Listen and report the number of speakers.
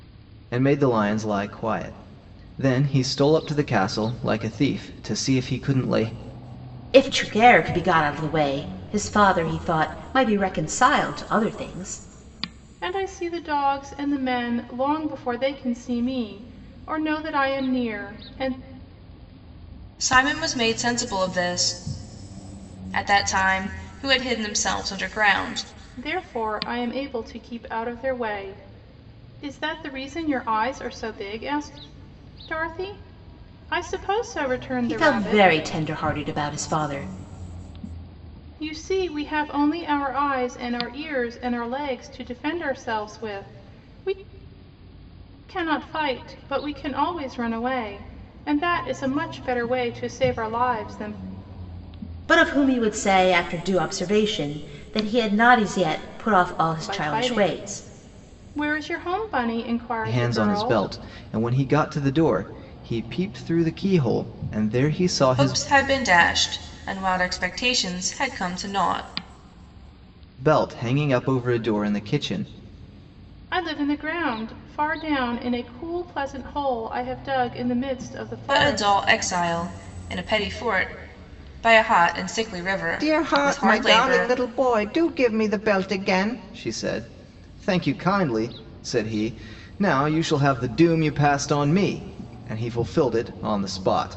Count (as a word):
four